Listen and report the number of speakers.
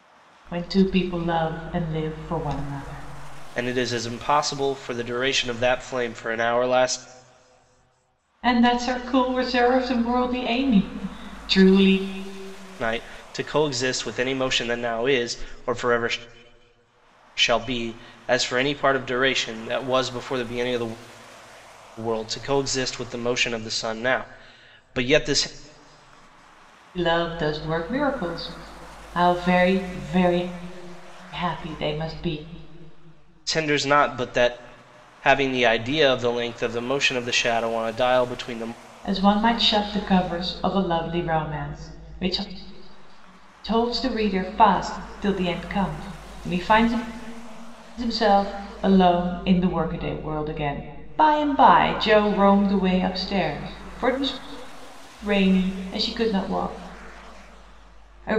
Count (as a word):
two